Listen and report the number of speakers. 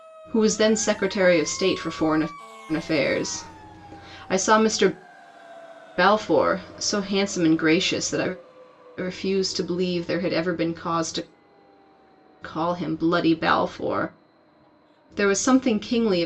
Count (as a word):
one